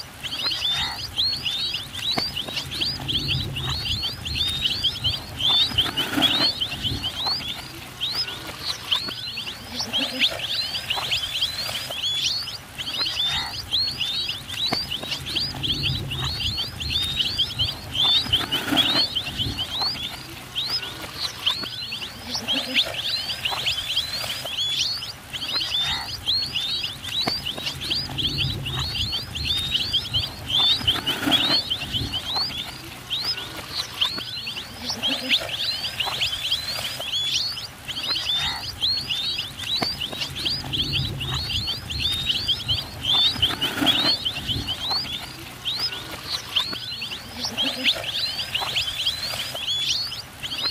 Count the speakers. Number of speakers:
0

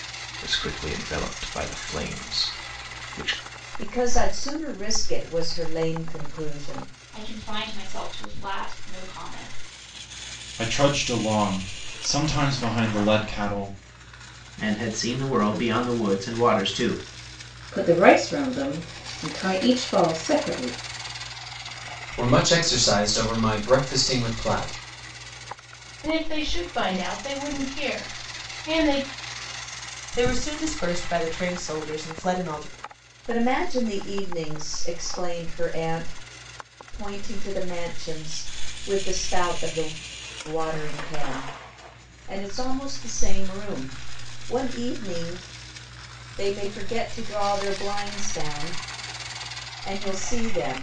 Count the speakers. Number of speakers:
9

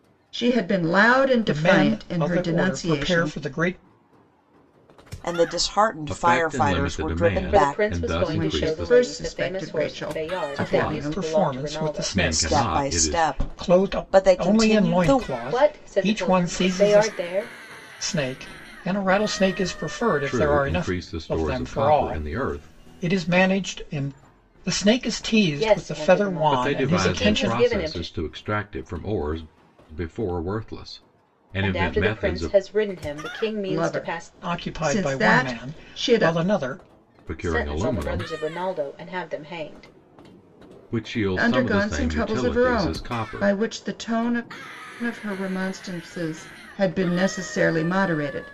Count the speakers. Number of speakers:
5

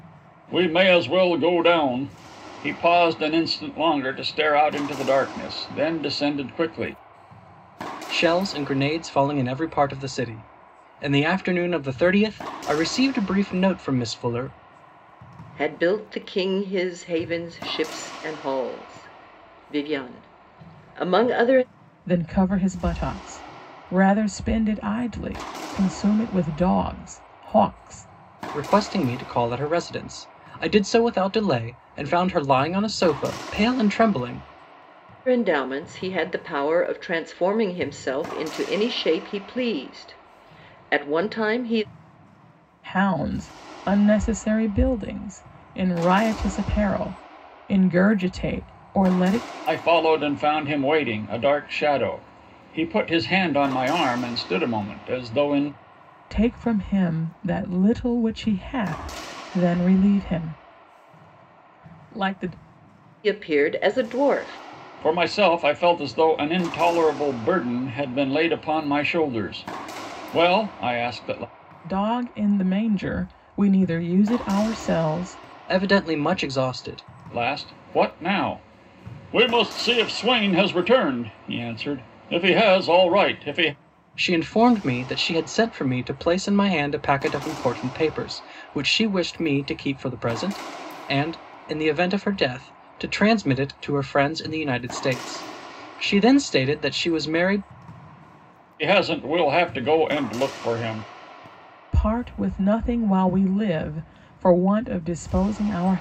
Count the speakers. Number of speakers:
4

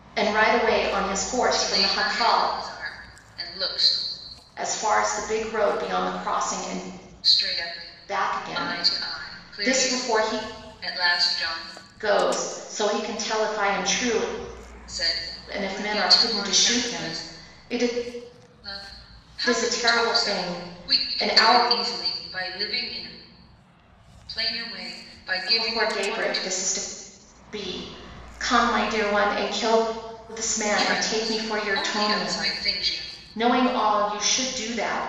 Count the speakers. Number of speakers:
2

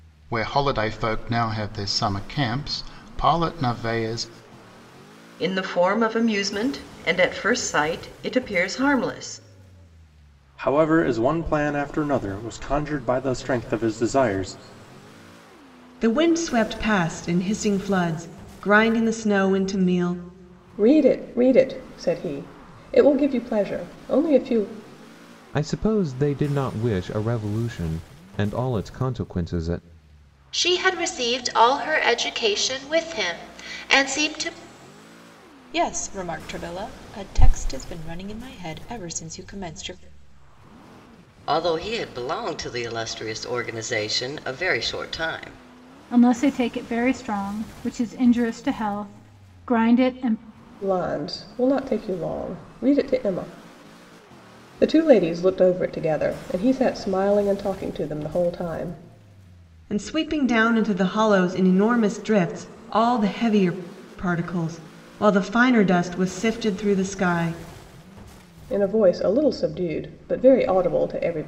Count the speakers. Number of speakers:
10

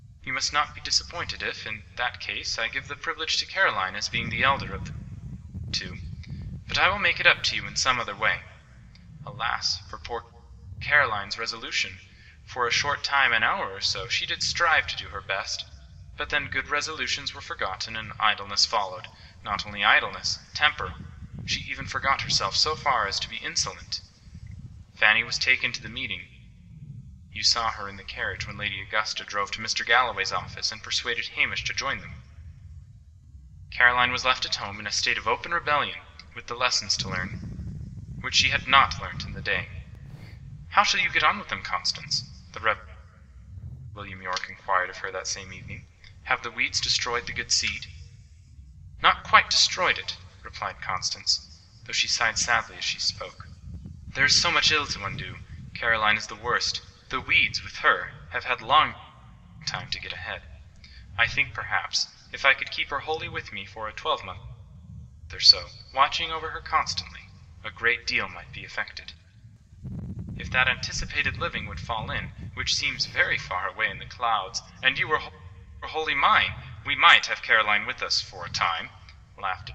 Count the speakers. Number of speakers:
1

